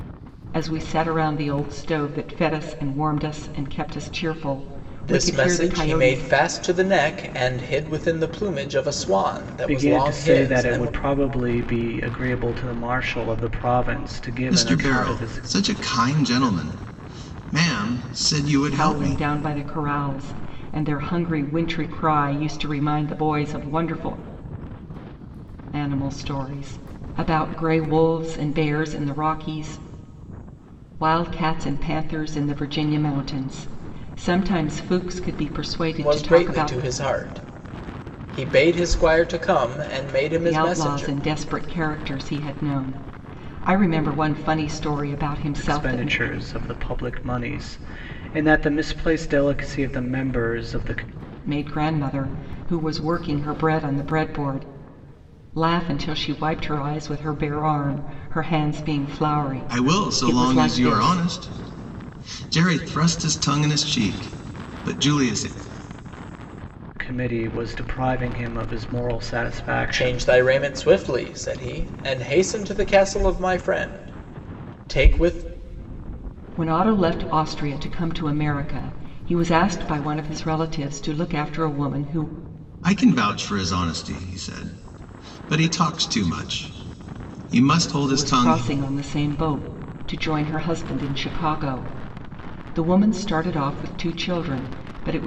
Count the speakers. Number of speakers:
4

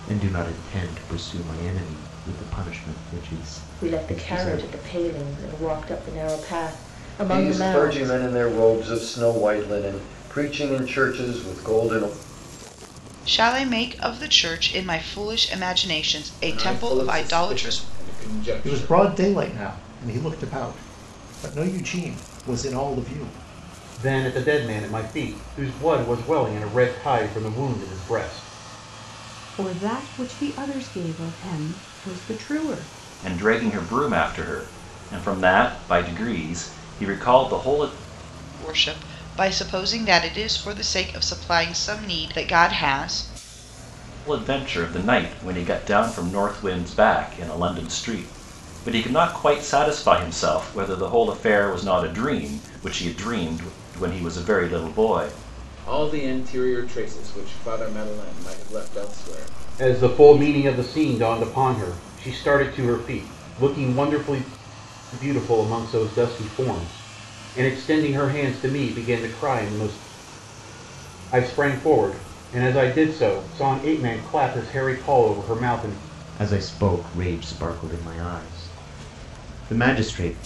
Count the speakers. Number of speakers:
9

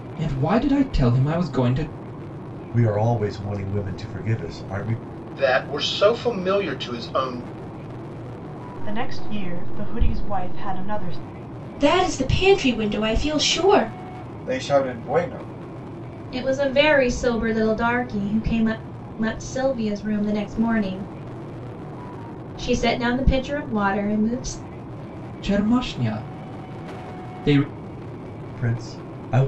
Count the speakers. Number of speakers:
7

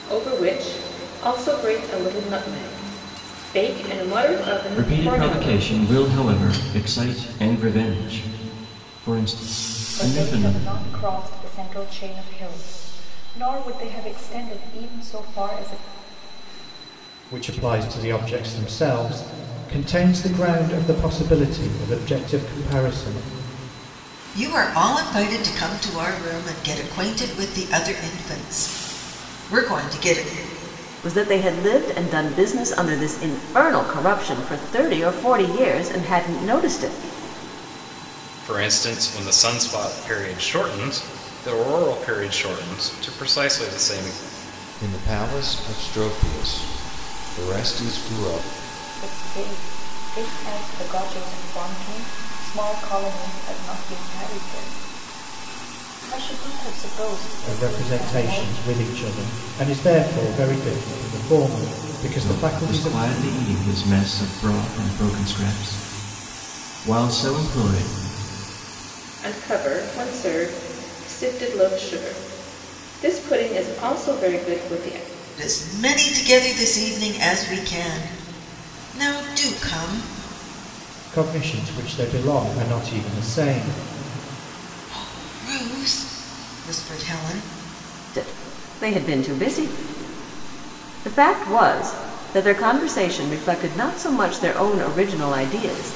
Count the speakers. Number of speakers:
8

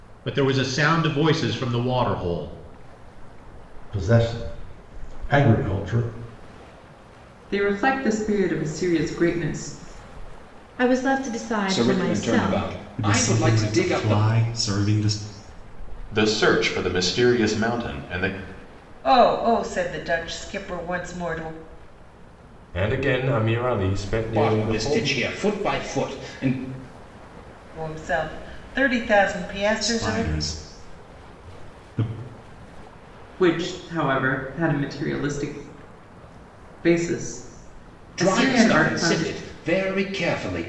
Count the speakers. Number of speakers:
9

